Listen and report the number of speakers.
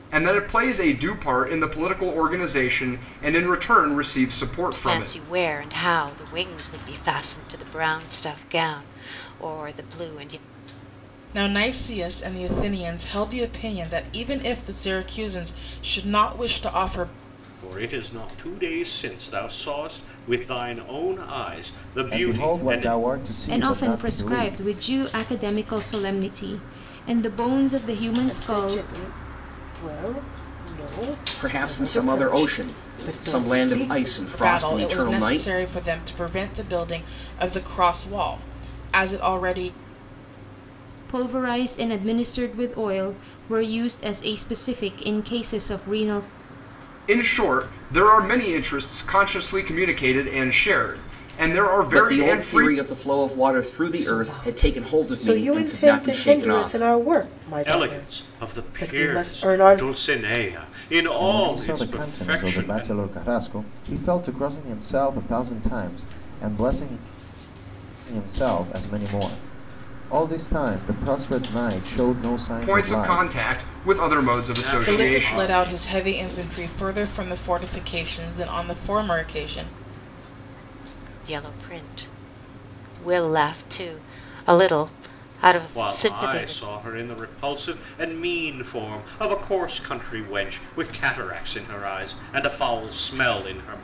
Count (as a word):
eight